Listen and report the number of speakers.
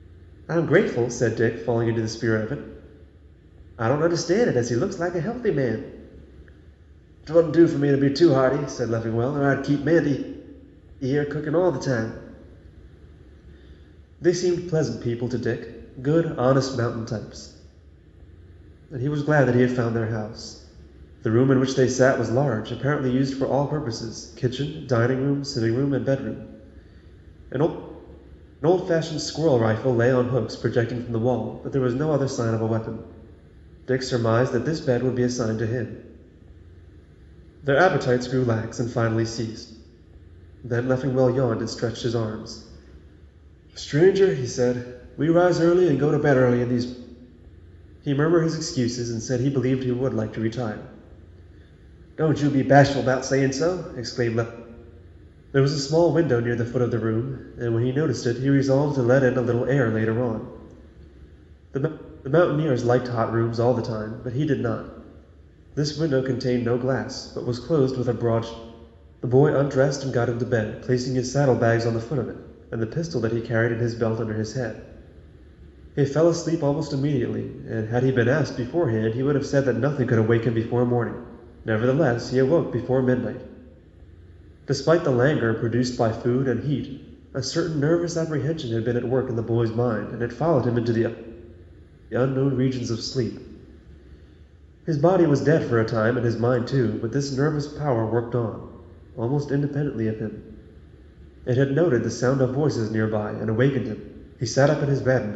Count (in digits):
1